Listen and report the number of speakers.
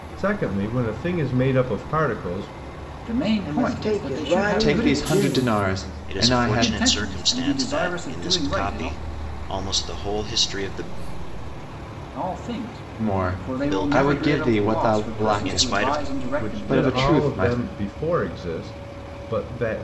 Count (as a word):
five